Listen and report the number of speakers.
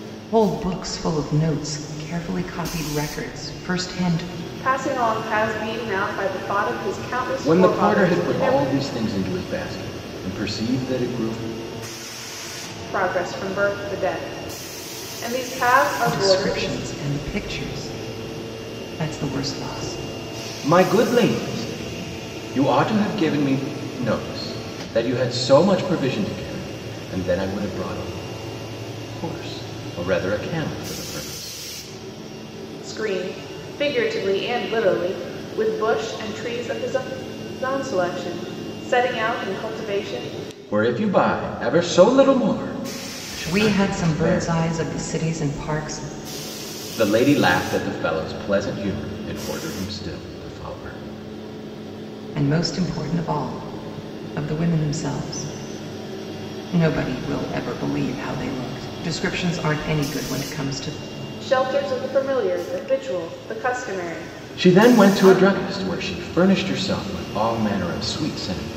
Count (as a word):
three